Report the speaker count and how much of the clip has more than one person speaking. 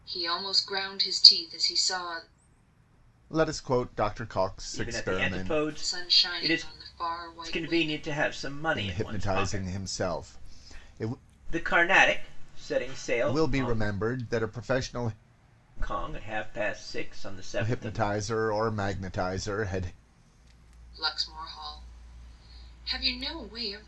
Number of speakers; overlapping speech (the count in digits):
3, about 19%